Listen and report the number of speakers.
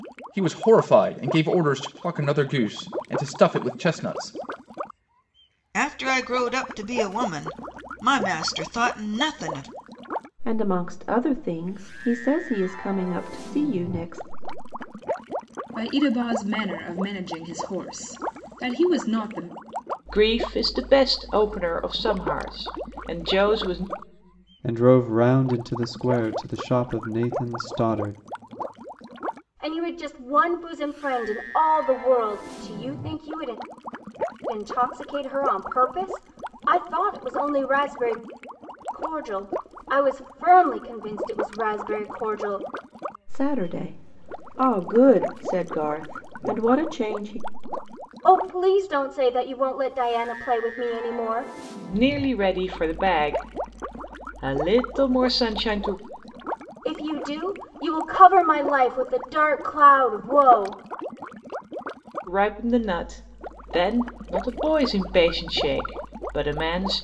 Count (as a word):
seven